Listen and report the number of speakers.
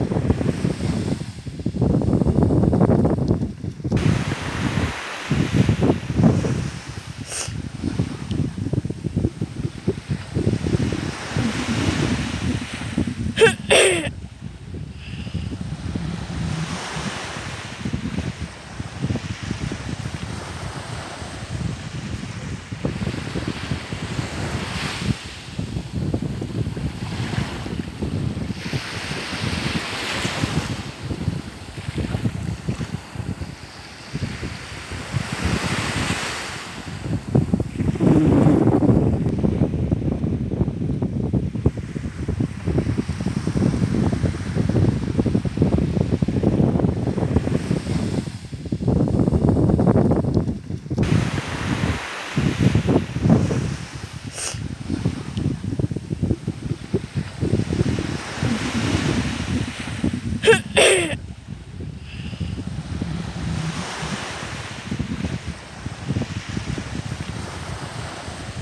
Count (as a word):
zero